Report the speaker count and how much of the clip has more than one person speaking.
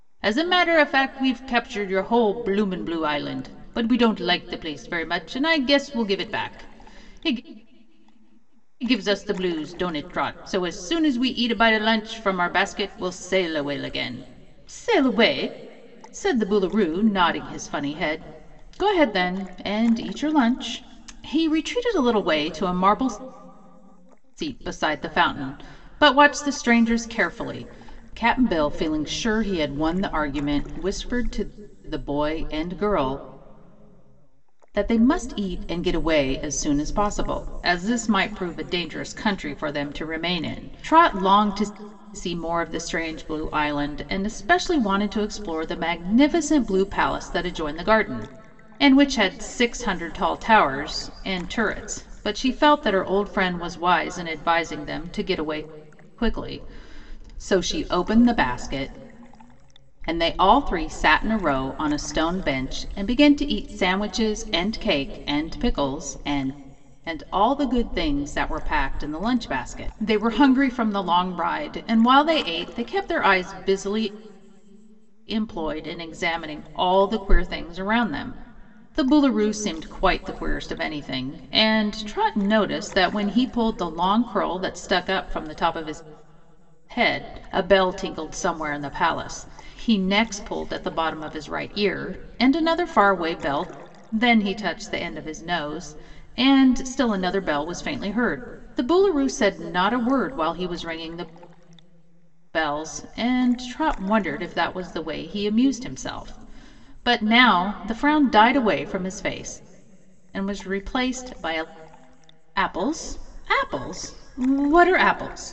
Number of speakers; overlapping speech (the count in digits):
1, no overlap